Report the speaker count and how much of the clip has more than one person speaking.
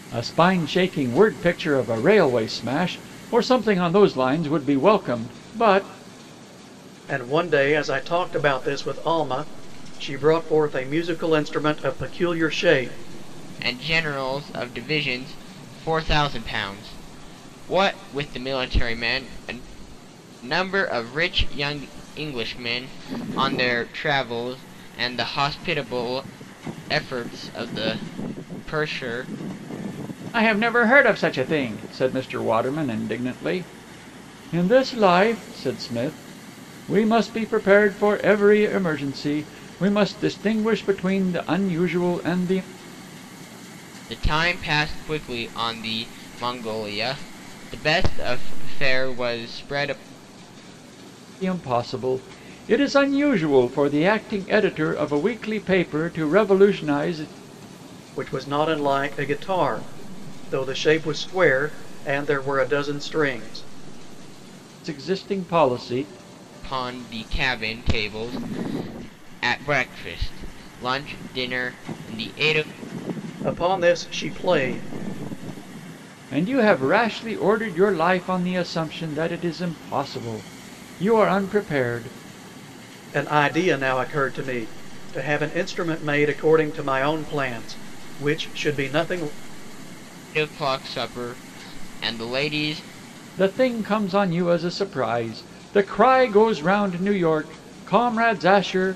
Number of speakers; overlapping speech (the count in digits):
3, no overlap